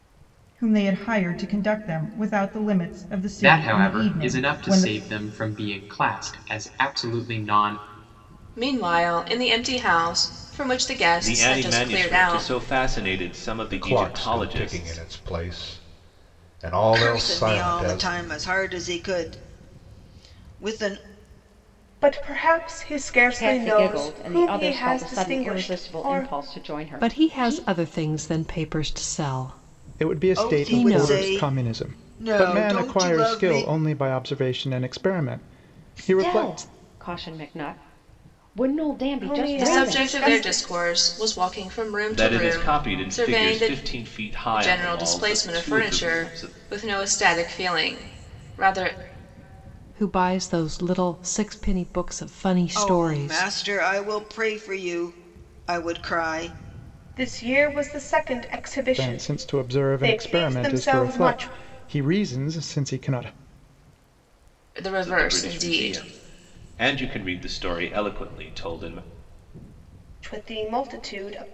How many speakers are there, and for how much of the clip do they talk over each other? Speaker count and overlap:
ten, about 32%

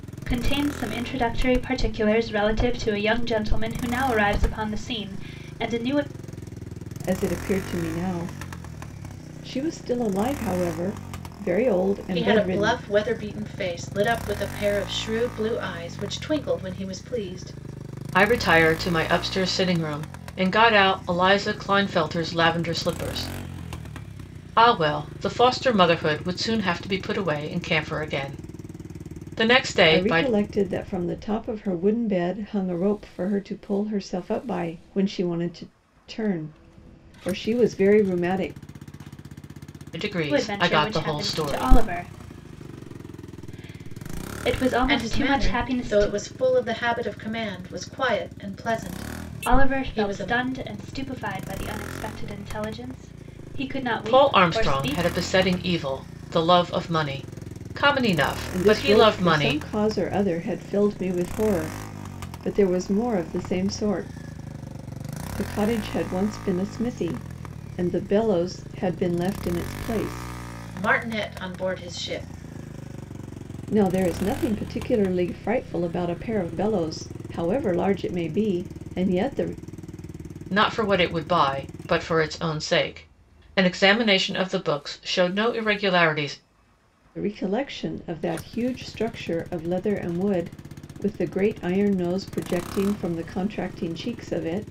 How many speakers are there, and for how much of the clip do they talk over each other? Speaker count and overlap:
four, about 8%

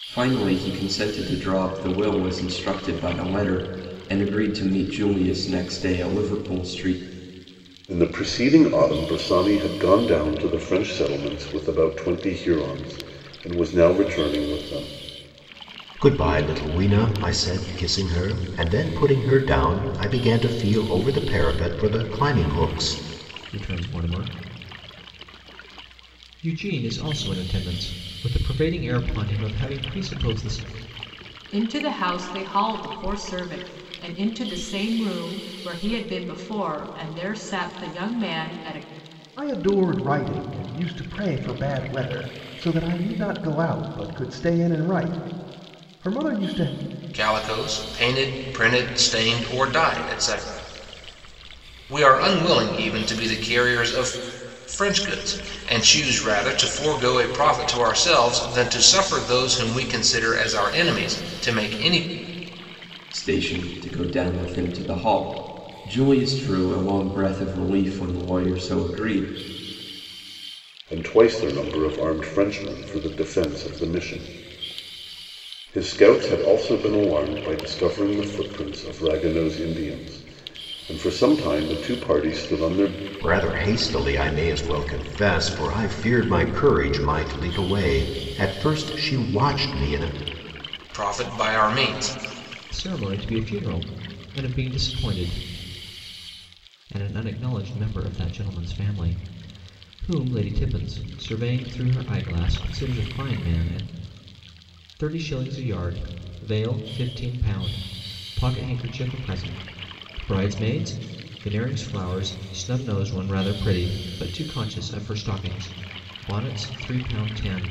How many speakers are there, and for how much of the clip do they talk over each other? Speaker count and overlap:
seven, no overlap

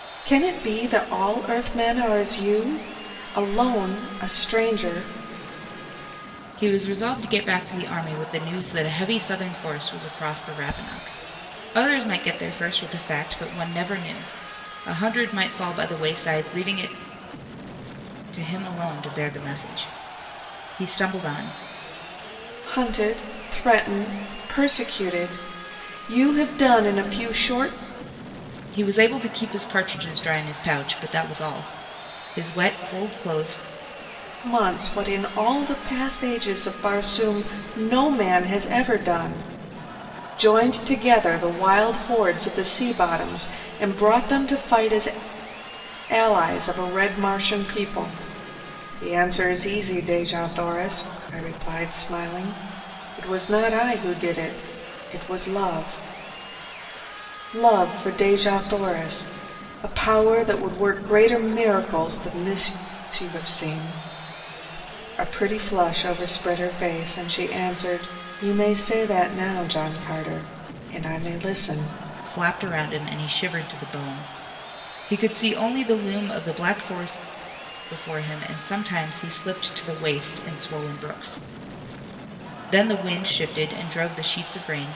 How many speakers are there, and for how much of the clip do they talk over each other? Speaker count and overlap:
two, no overlap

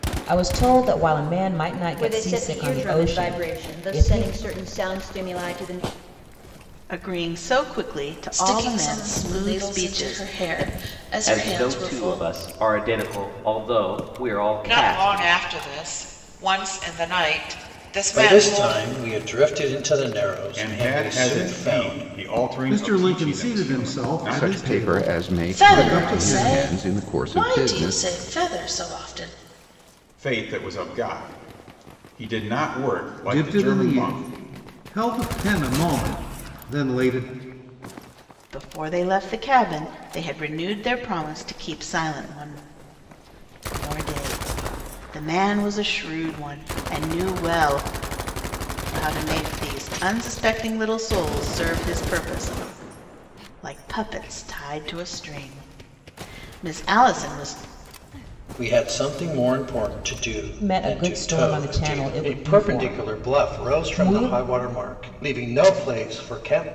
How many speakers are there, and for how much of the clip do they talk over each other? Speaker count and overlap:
ten, about 29%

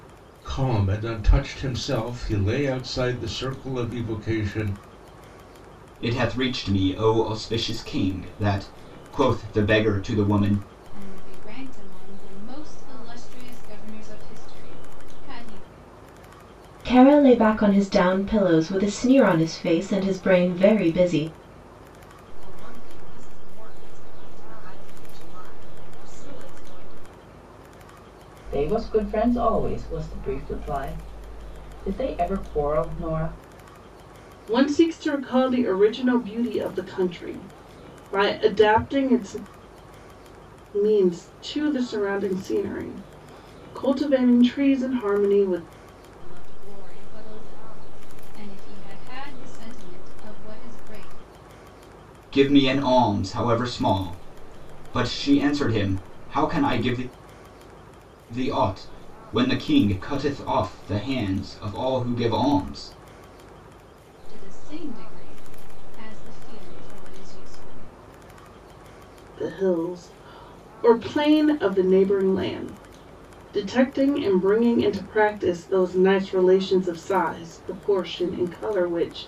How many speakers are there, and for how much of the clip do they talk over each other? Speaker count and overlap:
seven, no overlap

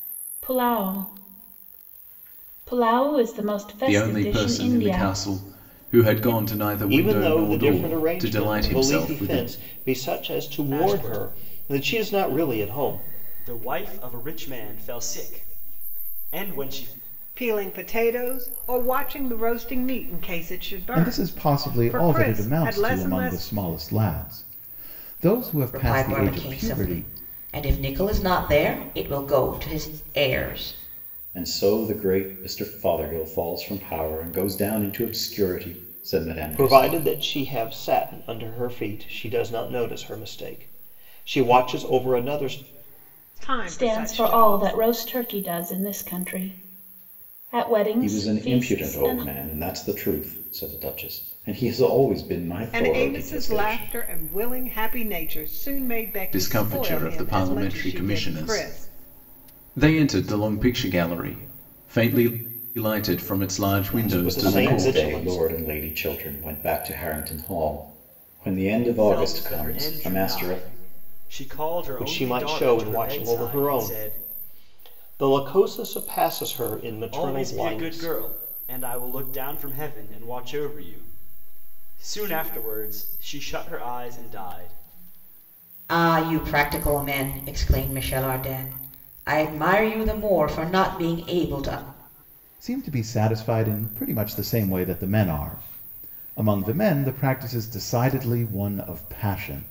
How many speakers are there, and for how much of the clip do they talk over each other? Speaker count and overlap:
eight, about 25%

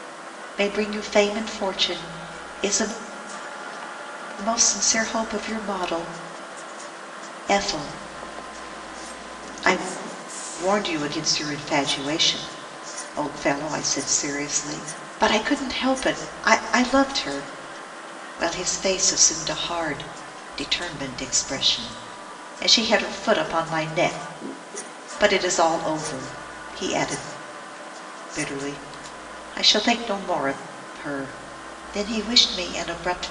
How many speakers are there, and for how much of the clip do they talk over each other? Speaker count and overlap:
one, no overlap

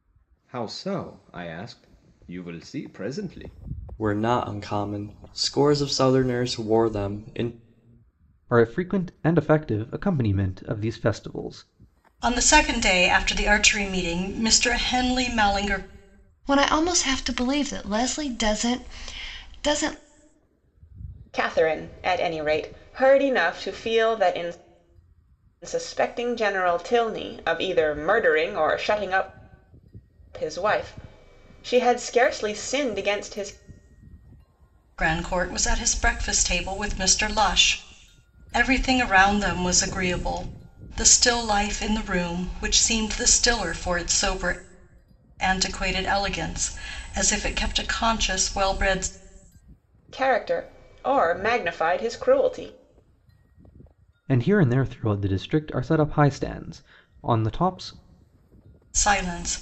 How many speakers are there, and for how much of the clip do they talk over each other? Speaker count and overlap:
six, no overlap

